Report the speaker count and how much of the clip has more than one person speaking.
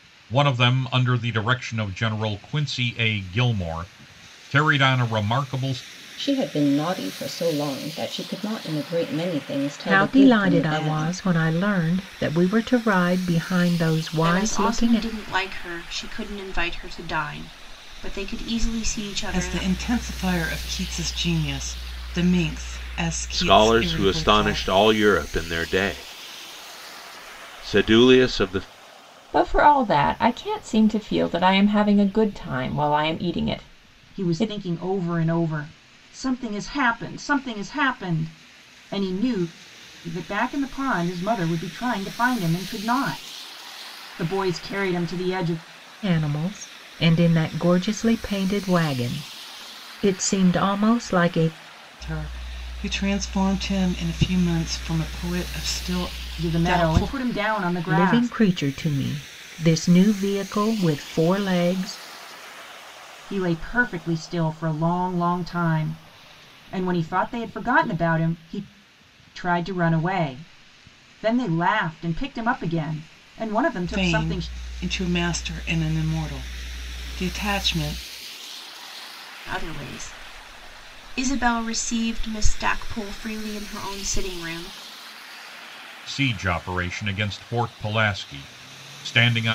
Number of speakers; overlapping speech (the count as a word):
eight, about 7%